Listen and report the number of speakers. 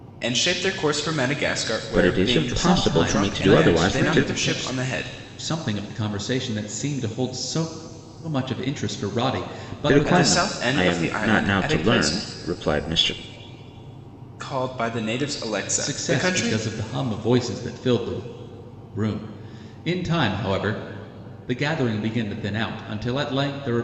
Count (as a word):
three